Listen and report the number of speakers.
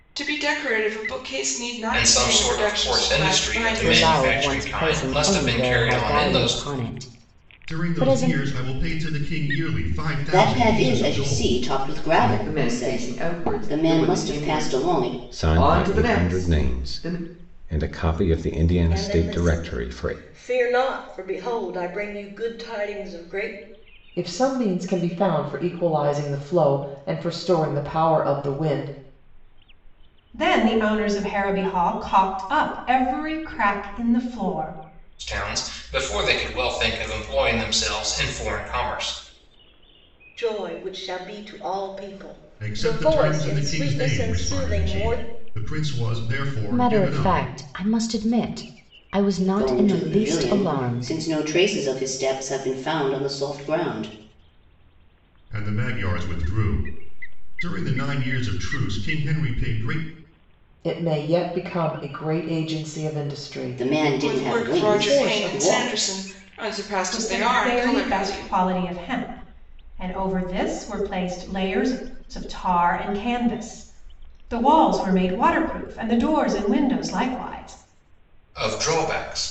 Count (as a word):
ten